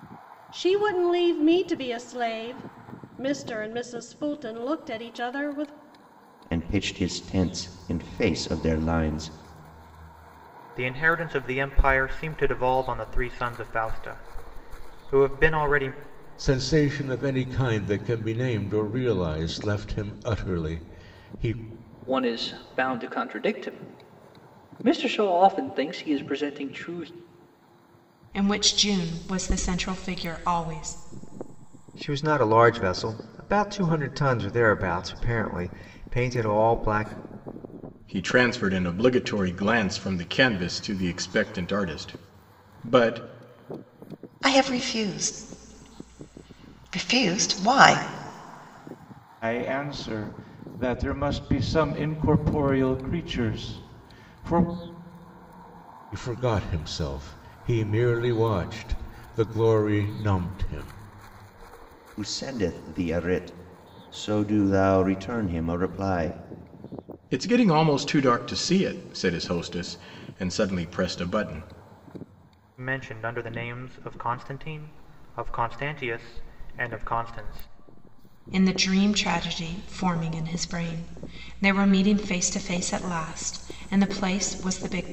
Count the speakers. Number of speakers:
10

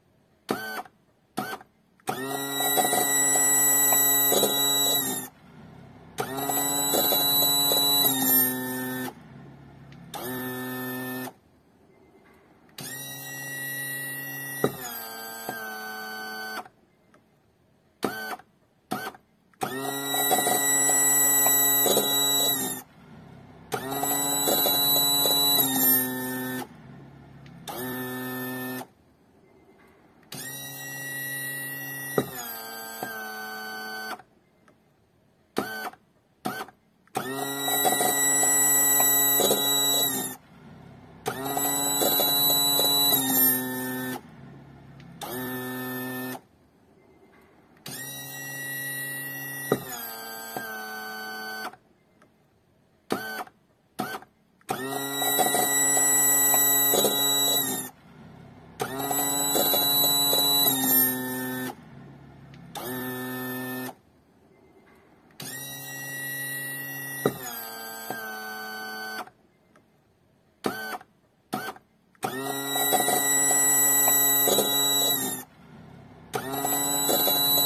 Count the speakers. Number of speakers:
0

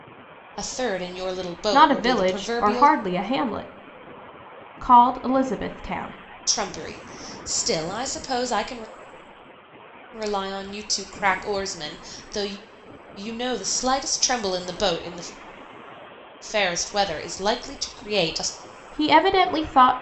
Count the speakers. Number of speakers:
2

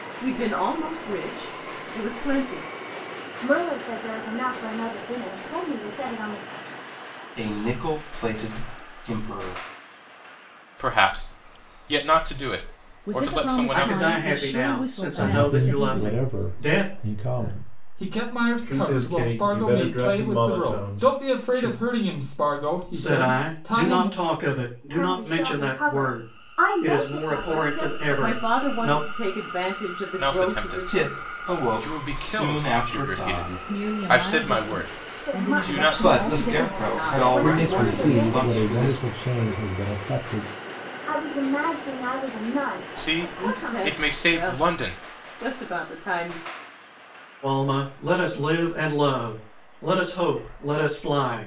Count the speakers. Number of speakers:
10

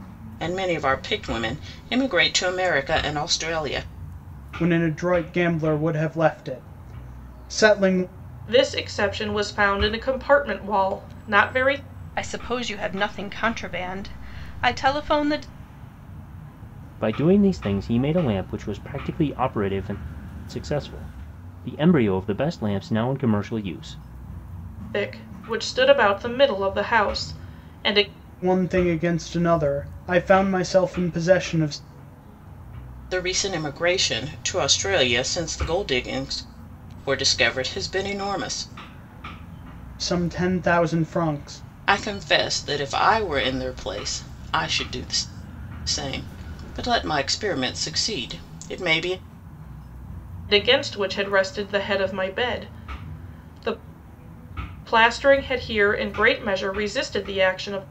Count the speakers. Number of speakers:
5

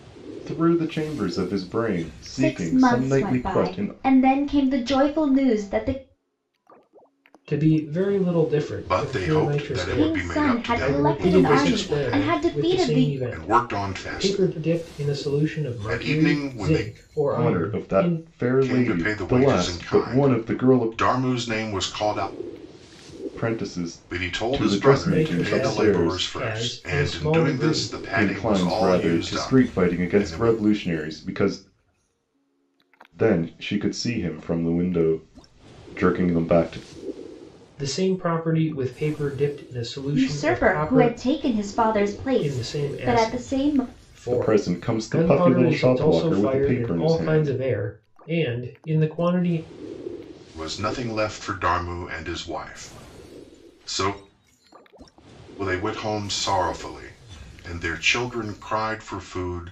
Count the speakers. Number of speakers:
4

